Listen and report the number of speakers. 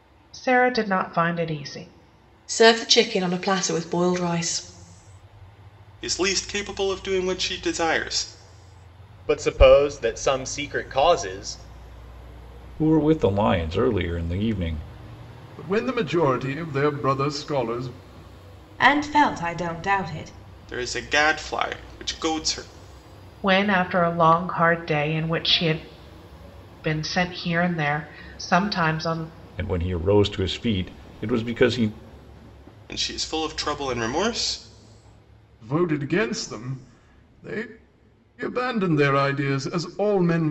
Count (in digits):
7